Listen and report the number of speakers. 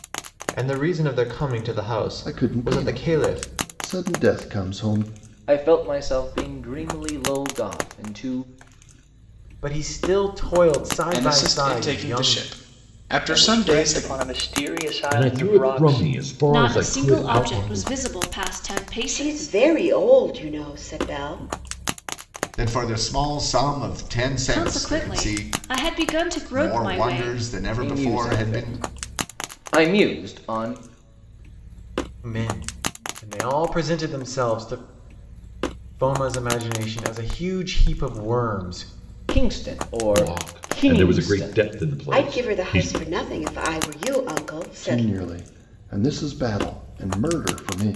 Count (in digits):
10